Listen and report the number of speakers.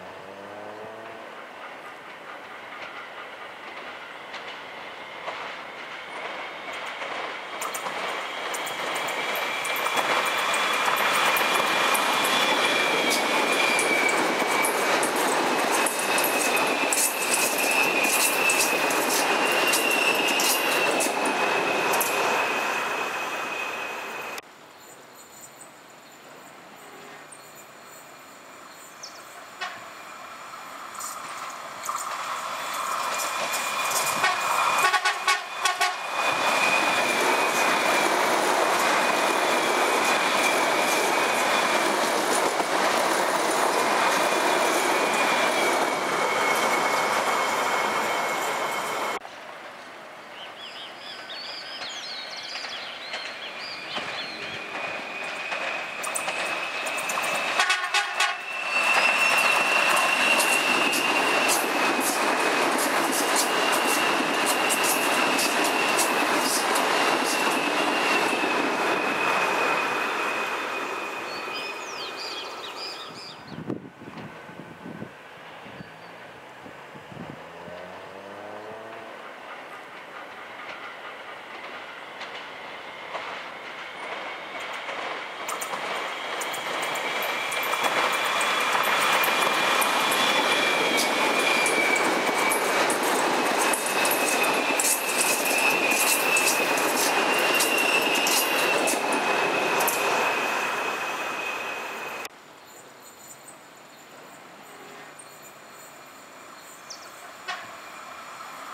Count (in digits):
0